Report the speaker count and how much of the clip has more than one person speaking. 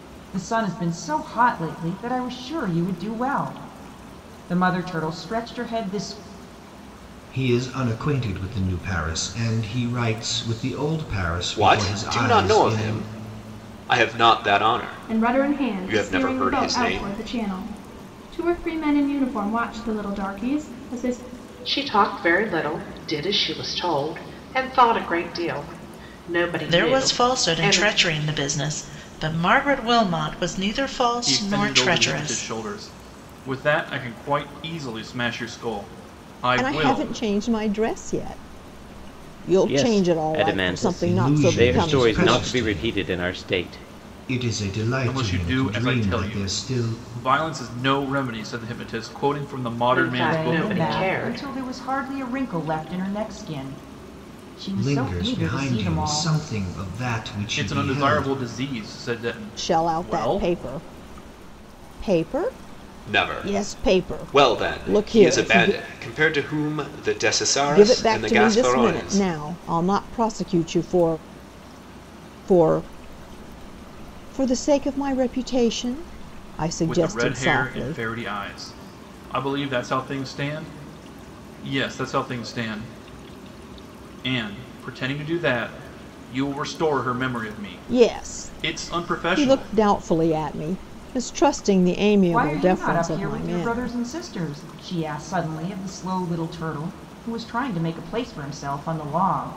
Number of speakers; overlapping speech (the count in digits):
9, about 27%